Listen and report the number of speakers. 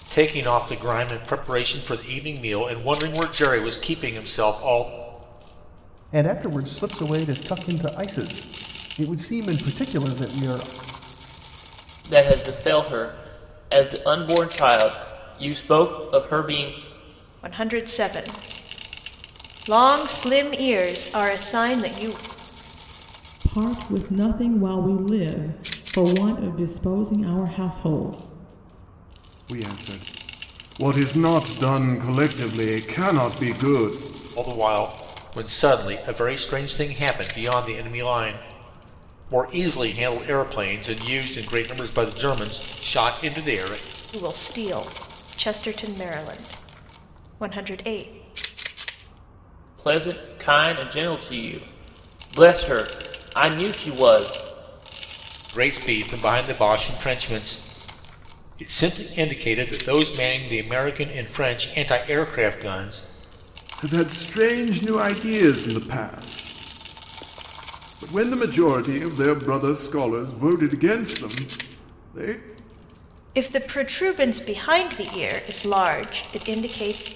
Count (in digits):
6